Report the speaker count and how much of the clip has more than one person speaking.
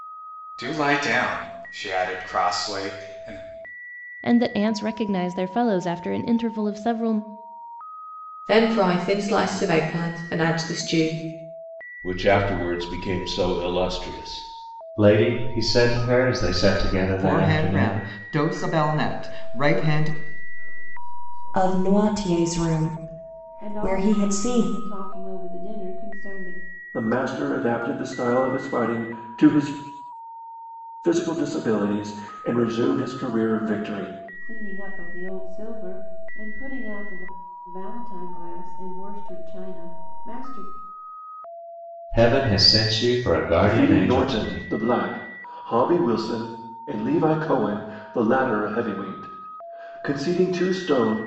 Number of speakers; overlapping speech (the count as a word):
ten, about 9%